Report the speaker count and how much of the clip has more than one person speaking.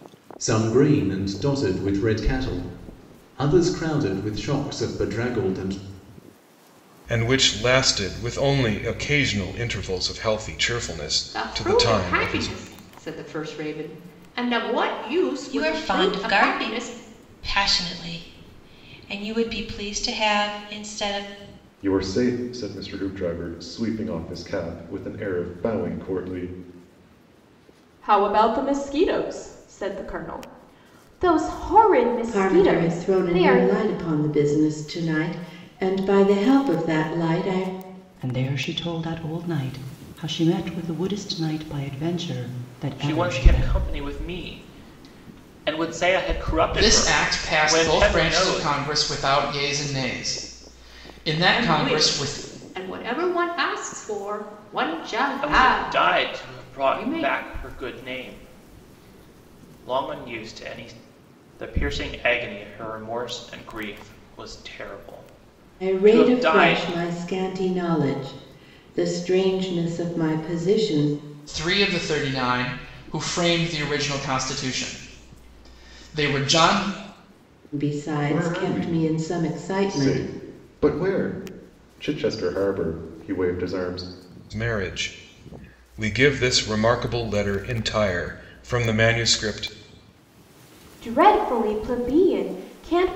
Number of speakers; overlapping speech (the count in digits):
10, about 14%